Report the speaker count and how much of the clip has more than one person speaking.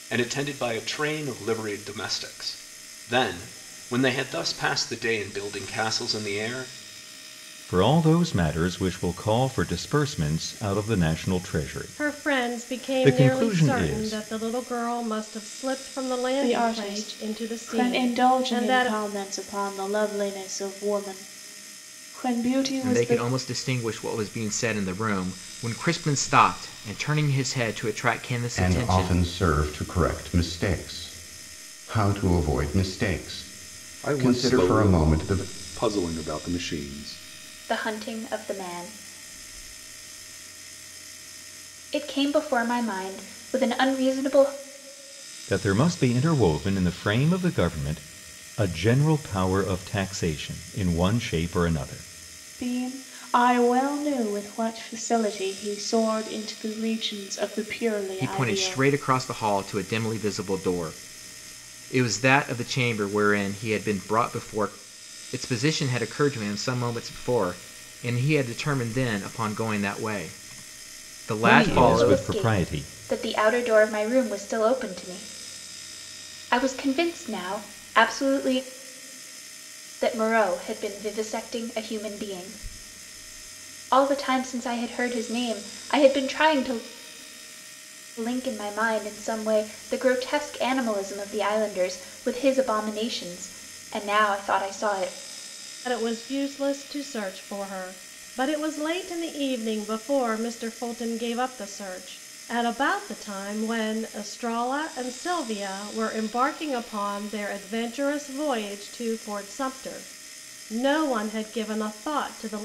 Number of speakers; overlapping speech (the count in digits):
8, about 9%